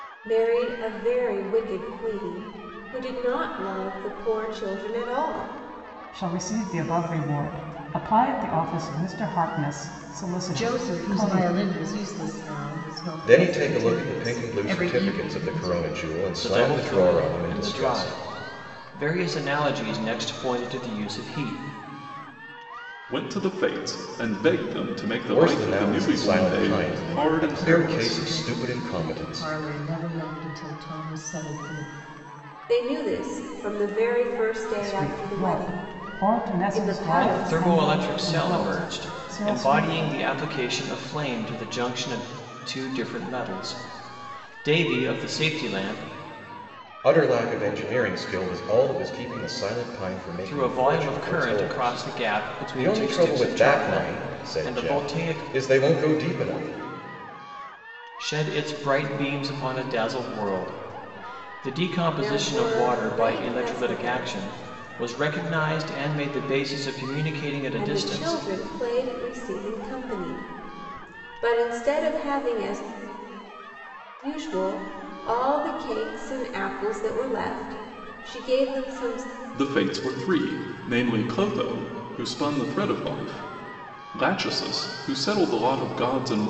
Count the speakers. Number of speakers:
6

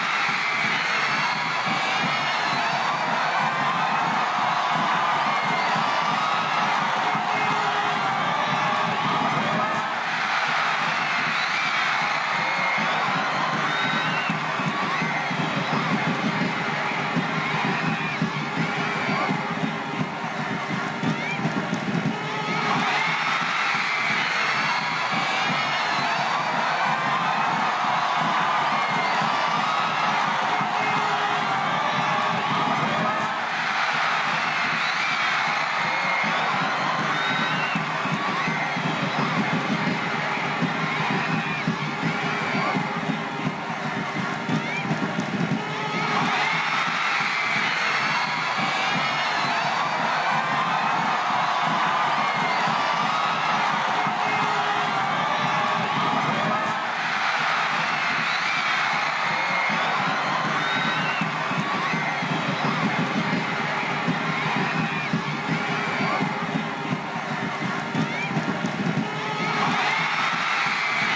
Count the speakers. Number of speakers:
0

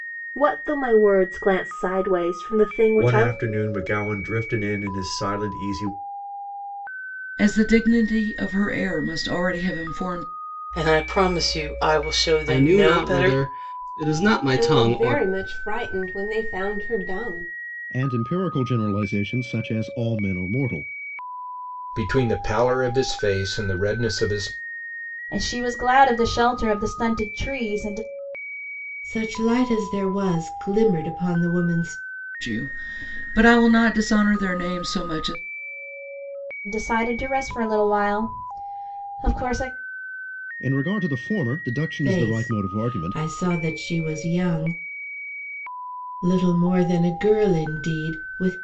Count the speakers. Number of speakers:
10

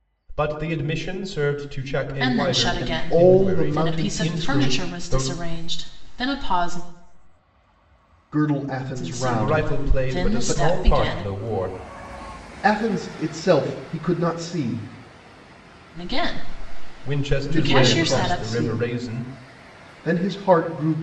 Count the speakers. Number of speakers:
3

